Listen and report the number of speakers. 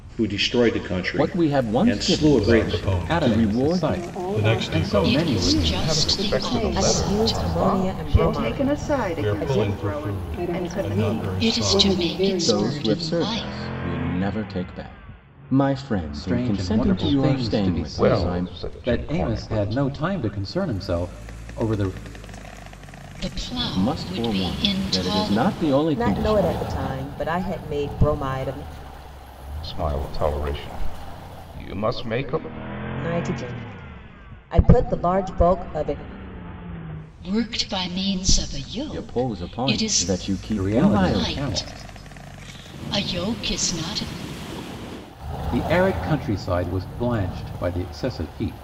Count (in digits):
9